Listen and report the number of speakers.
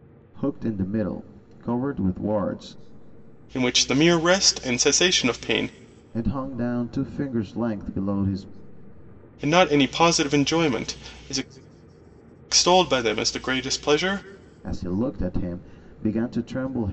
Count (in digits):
2